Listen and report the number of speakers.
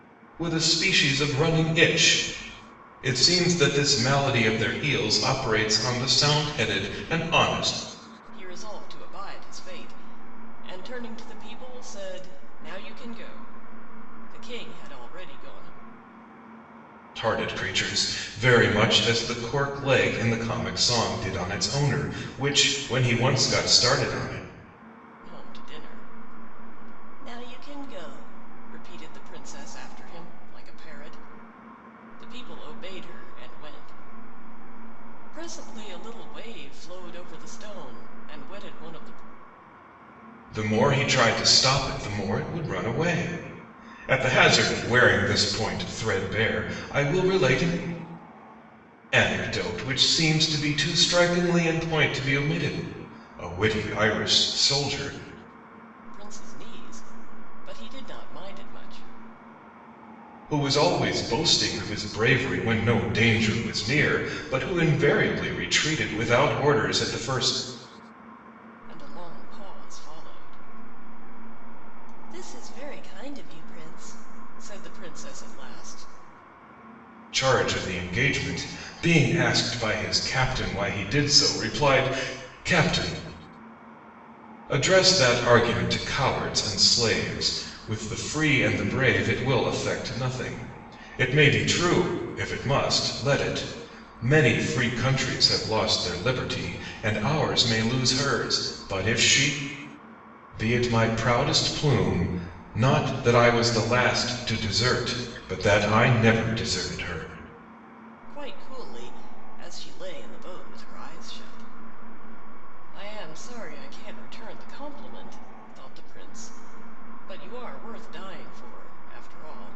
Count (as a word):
two